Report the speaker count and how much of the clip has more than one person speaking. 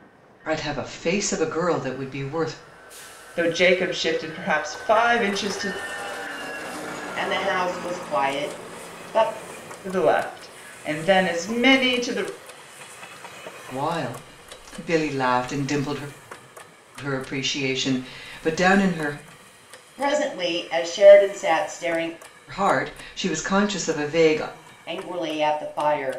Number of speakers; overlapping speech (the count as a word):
three, no overlap